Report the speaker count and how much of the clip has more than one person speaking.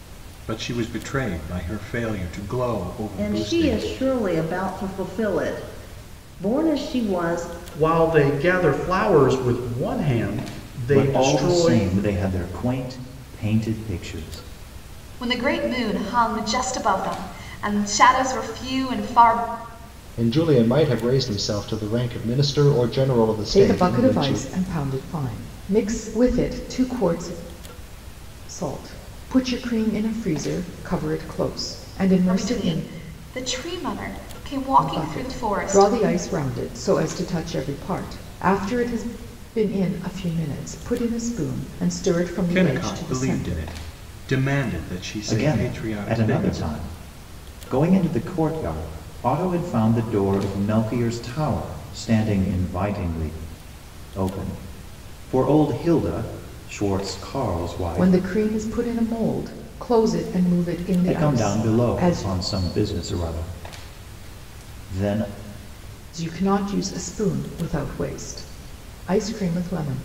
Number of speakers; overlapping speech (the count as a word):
seven, about 12%